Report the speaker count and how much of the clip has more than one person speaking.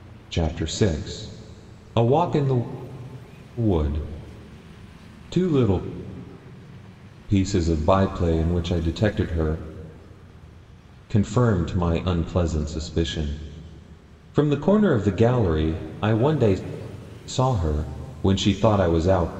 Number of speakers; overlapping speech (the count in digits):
1, no overlap